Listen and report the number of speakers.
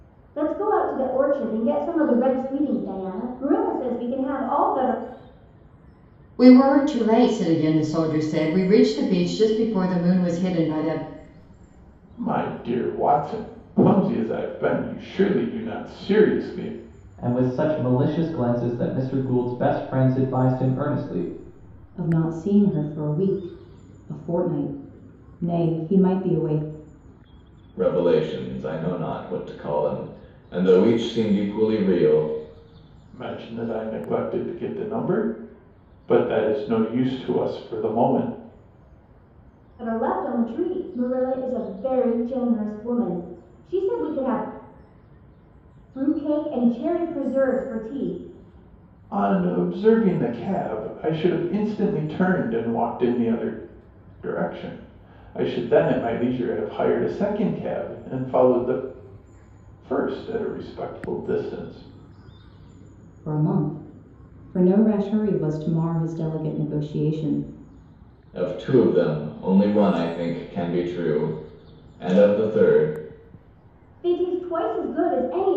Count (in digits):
6